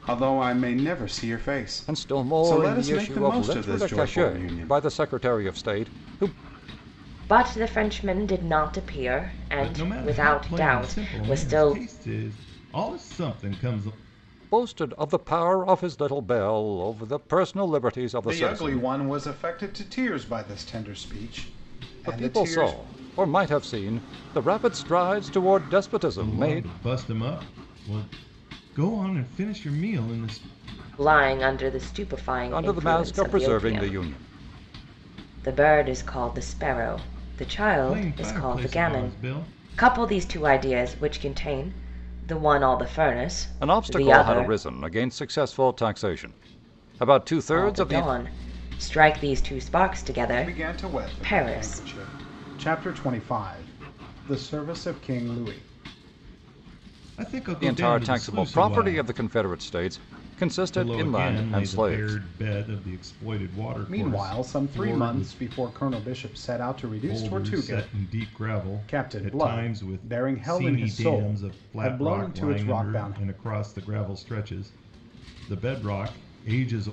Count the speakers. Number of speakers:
4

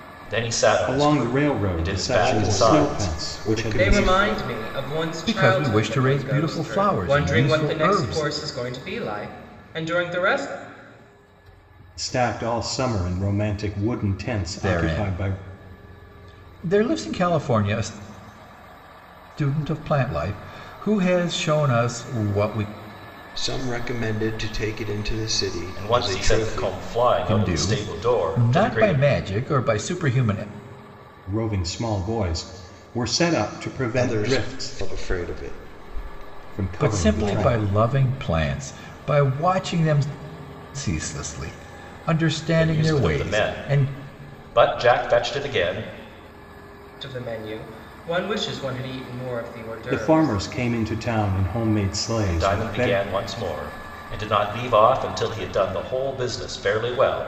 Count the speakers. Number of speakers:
5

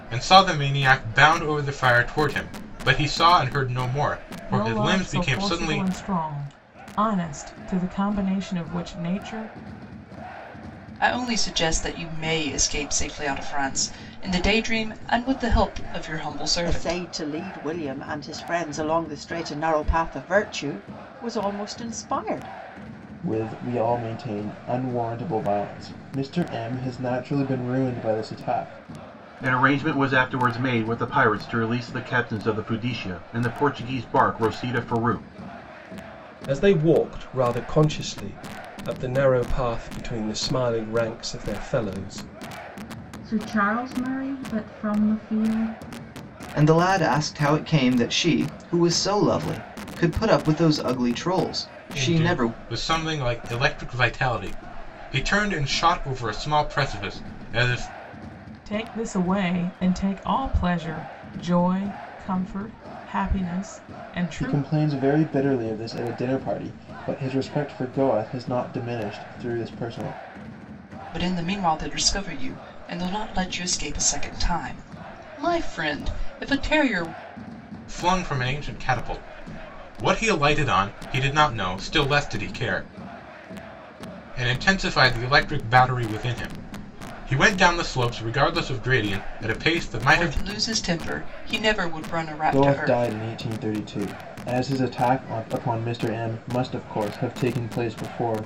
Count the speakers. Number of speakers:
9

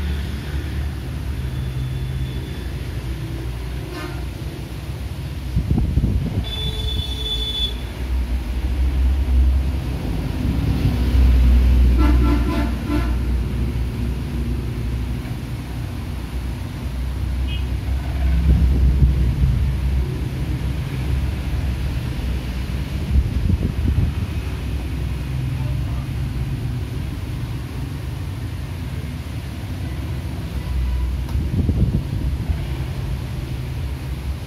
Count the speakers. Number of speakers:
0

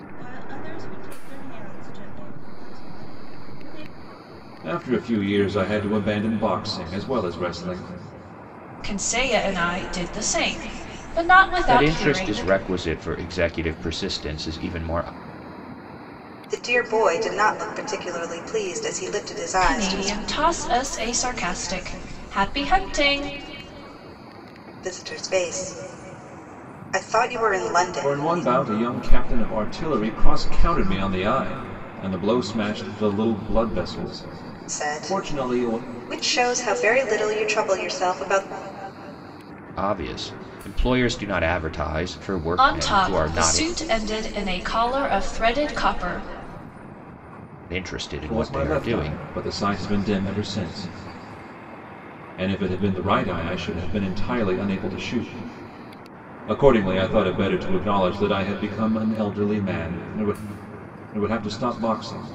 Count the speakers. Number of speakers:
5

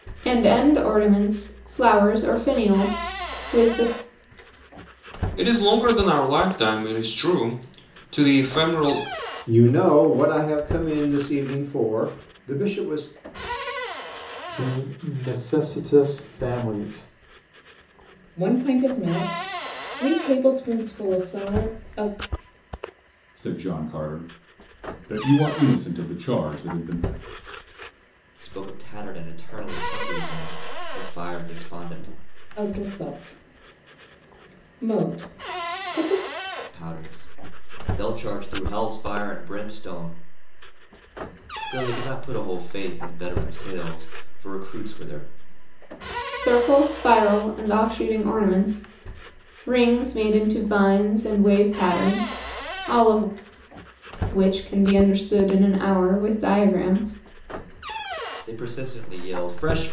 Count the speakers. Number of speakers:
7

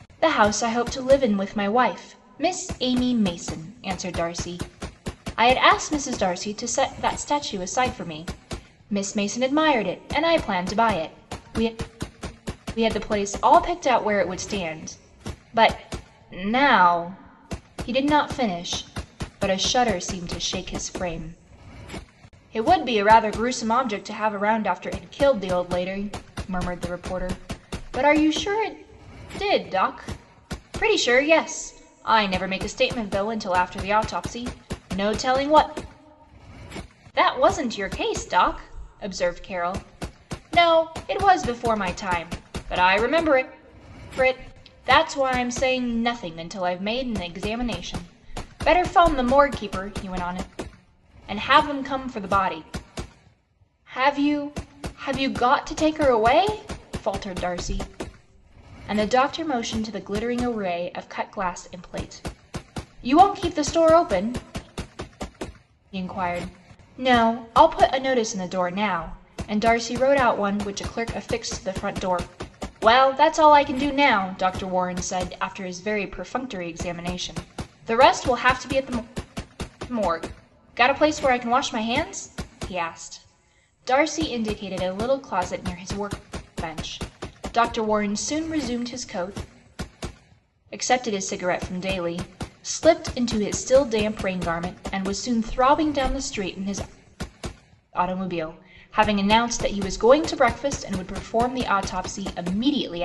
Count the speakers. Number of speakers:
1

